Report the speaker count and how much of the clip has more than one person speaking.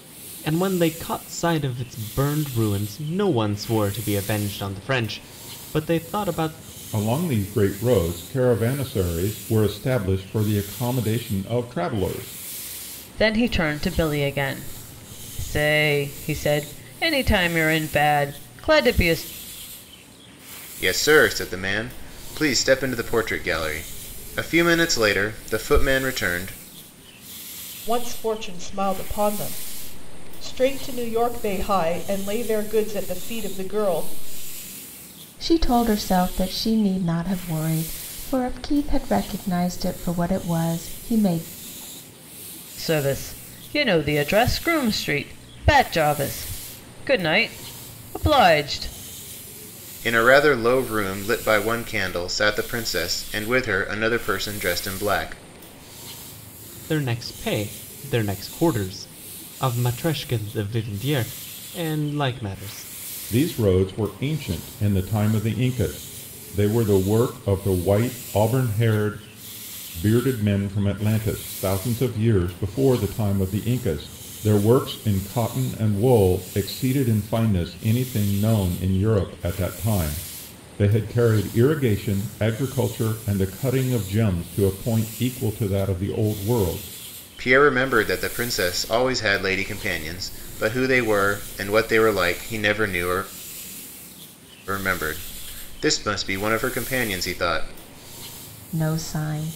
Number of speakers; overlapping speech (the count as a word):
six, no overlap